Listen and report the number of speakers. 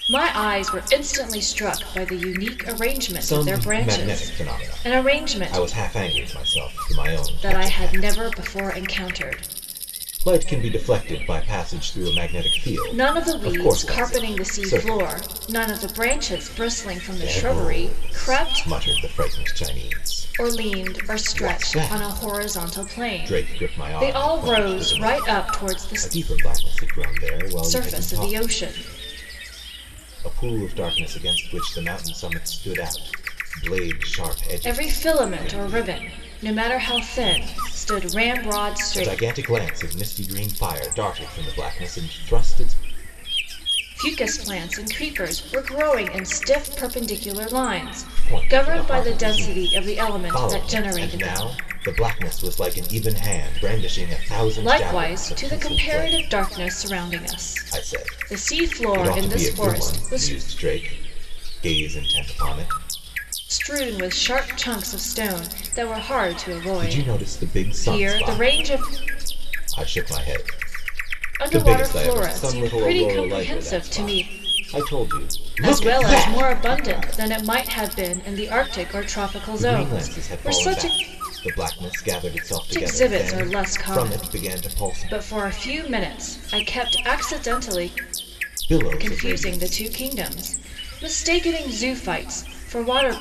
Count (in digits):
2